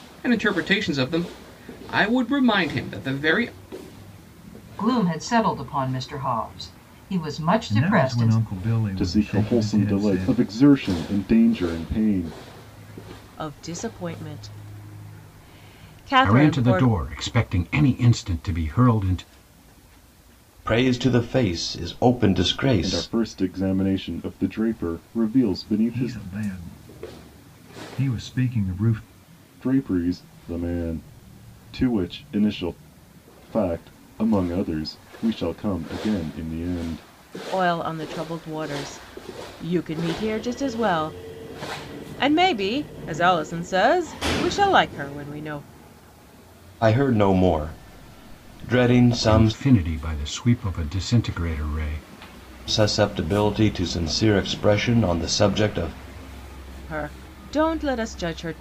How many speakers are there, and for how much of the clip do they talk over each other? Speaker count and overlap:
7, about 7%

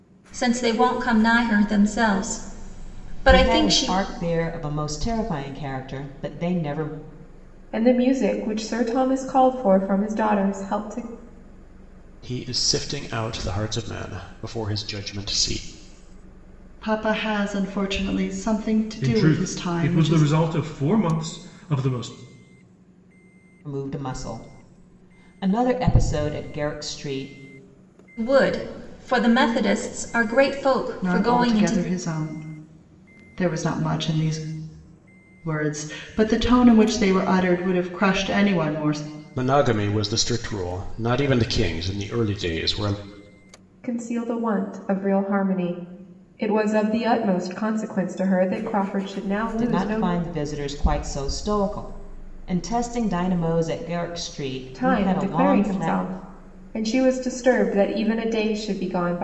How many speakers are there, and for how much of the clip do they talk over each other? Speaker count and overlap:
6, about 8%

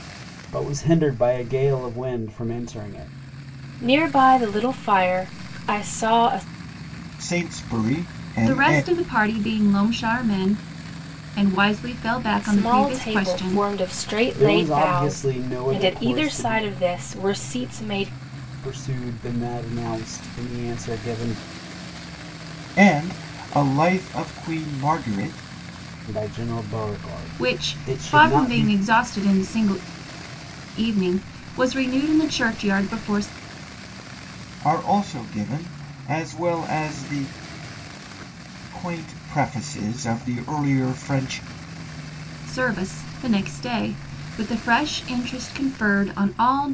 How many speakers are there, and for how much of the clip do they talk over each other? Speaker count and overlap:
4, about 11%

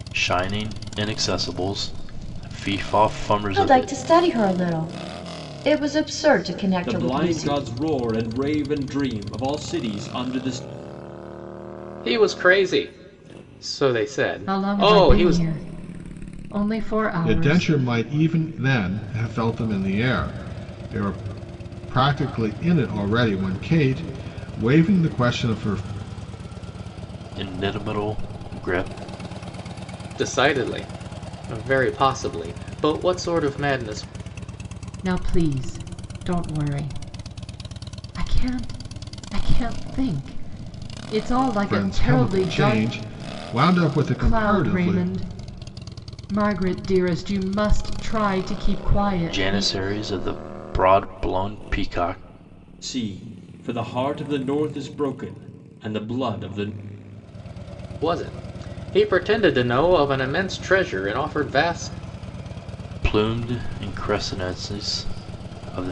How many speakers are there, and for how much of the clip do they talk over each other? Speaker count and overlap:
6, about 8%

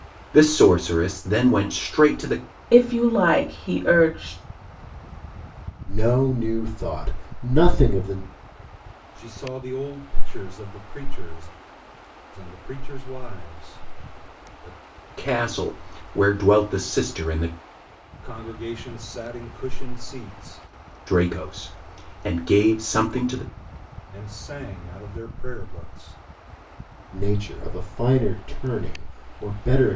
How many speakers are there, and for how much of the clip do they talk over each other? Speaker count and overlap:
4, no overlap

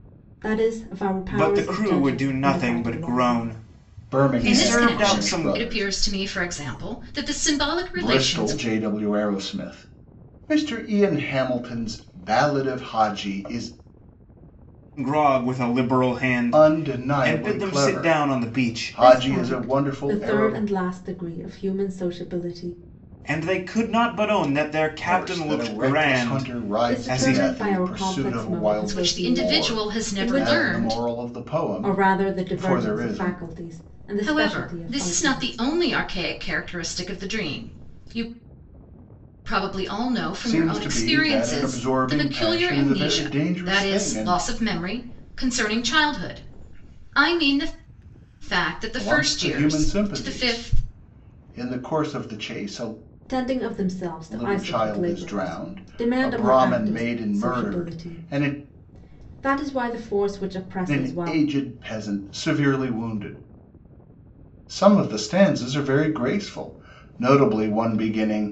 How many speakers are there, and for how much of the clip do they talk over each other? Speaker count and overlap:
4, about 41%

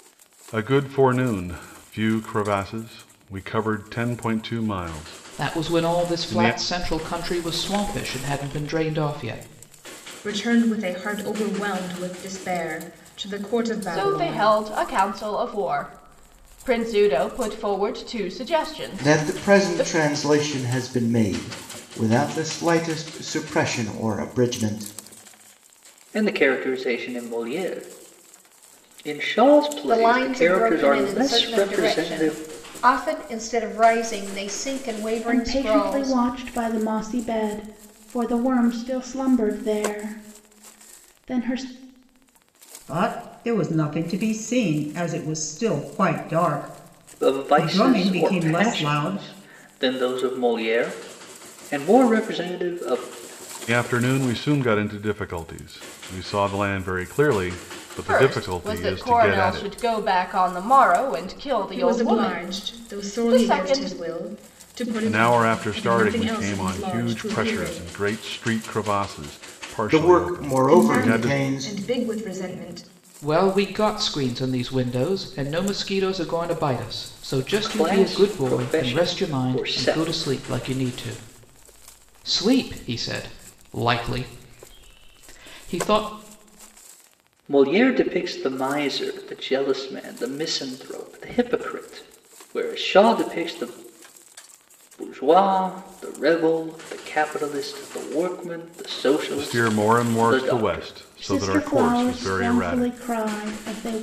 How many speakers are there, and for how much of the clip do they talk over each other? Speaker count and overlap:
9, about 23%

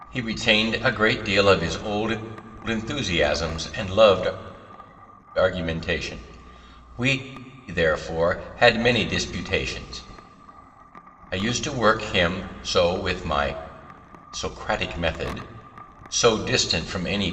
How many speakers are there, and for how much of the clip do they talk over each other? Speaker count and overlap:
1, no overlap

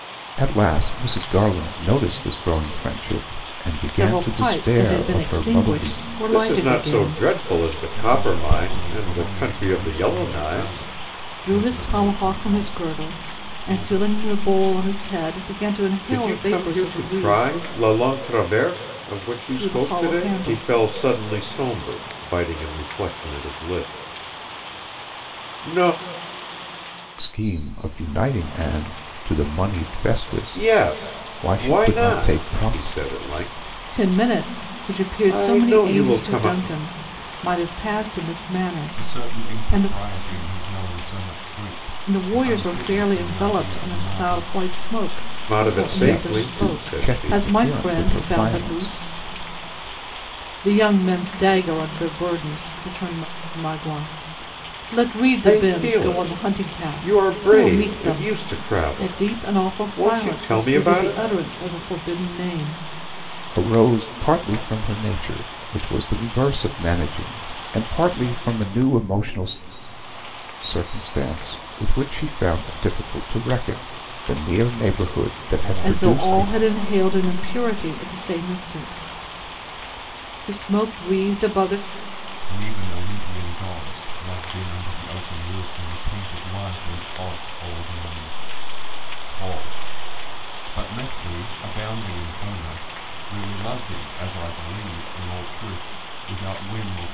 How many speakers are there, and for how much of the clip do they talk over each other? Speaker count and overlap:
4, about 31%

